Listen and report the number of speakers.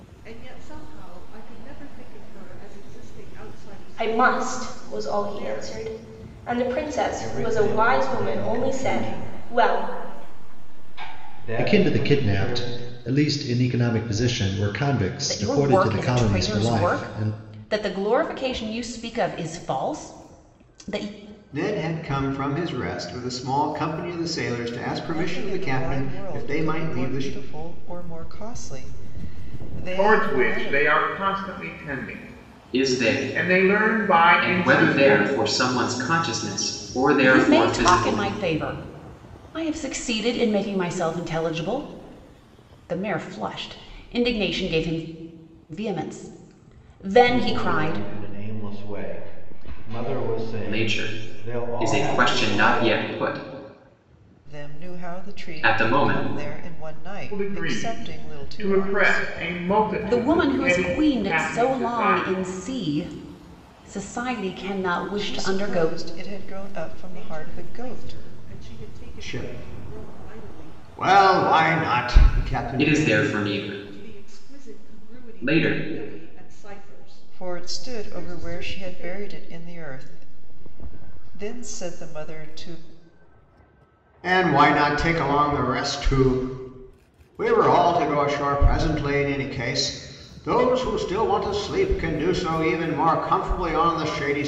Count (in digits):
9